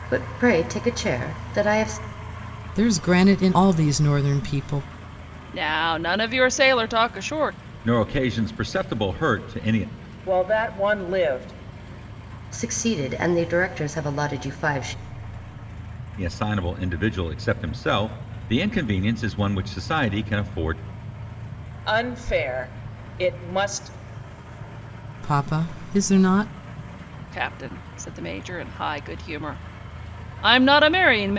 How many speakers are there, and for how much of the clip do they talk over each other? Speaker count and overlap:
5, no overlap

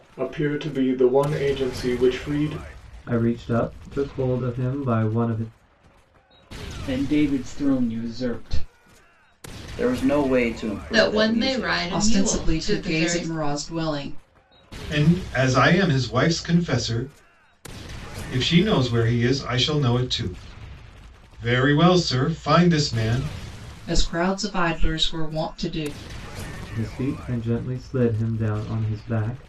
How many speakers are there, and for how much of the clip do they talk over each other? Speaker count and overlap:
7, about 8%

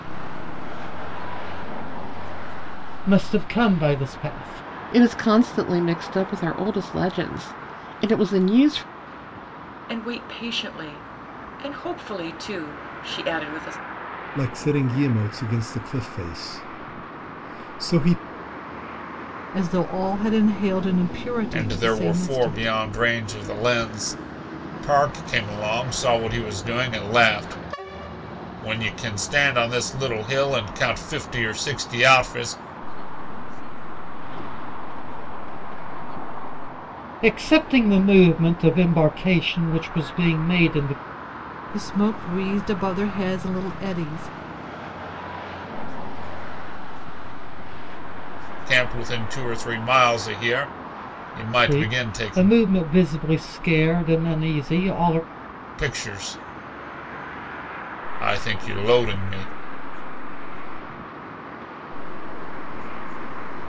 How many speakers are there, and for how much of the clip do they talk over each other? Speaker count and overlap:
7, about 8%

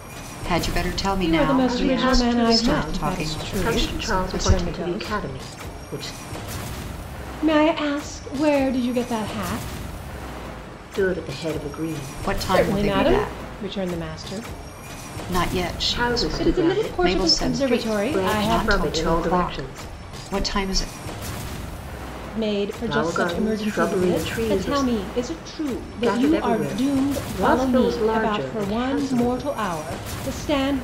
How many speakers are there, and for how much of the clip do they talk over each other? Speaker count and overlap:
3, about 48%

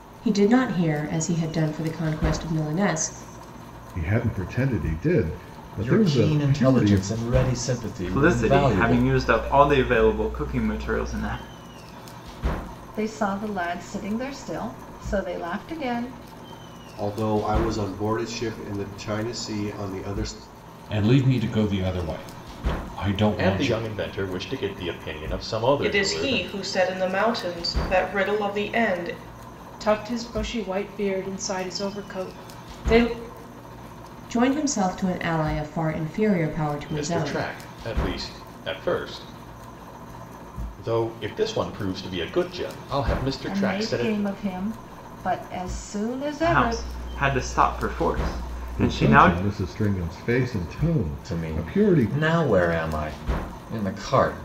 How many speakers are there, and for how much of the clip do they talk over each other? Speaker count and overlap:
10, about 12%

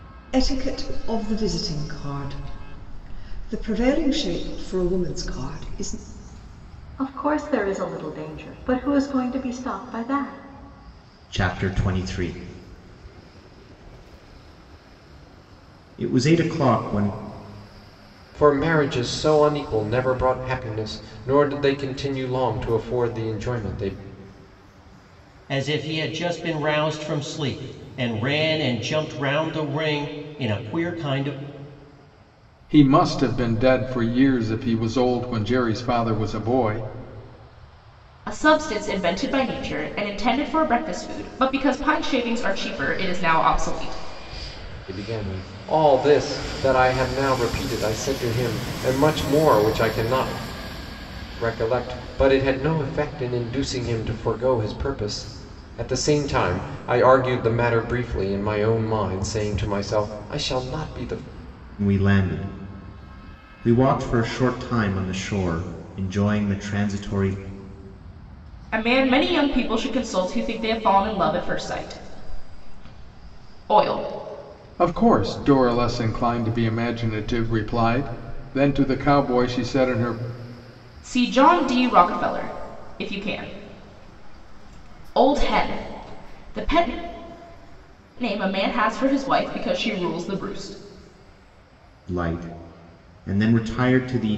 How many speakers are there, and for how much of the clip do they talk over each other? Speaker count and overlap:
7, no overlap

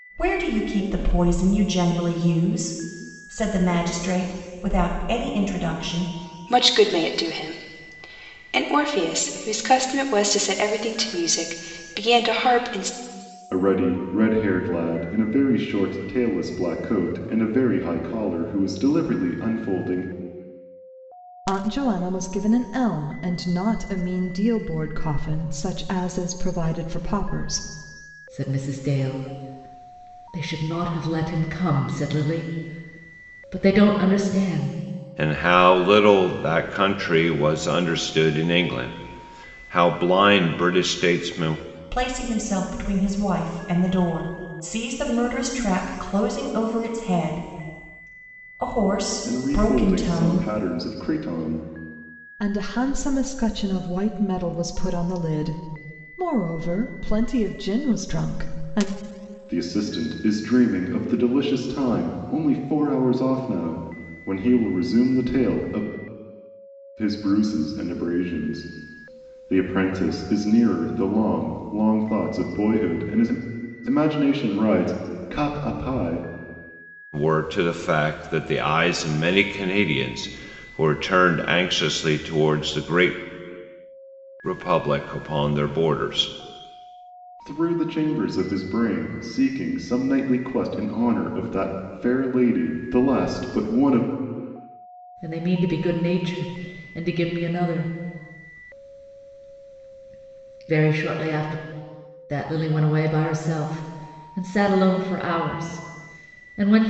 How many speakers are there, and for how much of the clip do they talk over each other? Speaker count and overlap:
6, about 1%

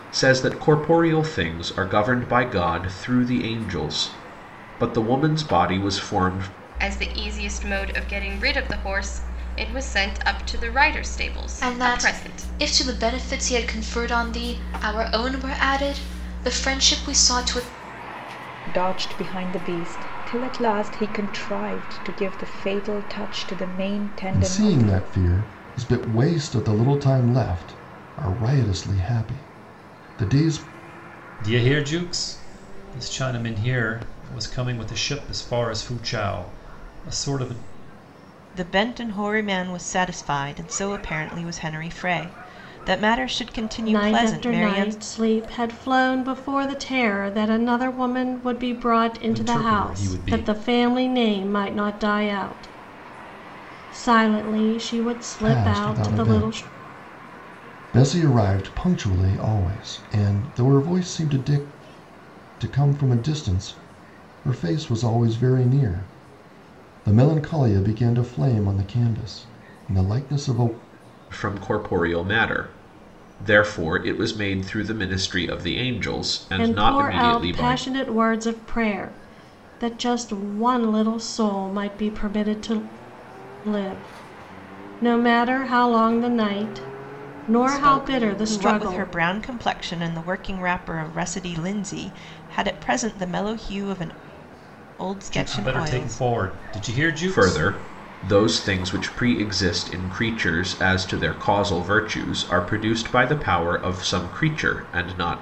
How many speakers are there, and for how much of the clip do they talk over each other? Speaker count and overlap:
8, about 9%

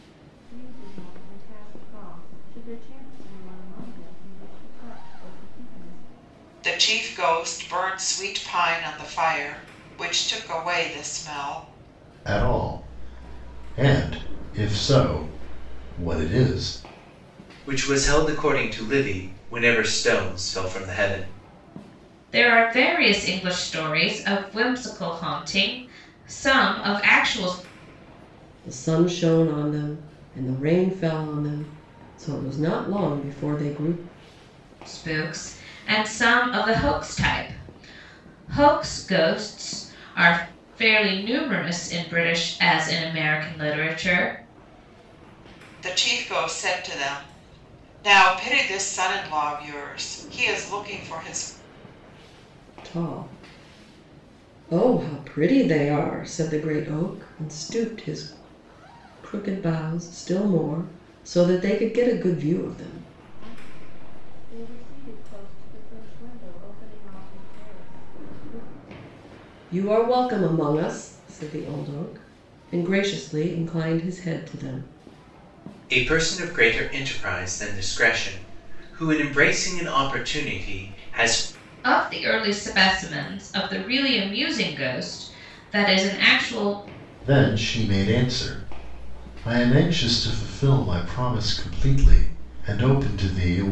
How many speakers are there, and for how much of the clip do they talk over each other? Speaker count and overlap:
6, no overlap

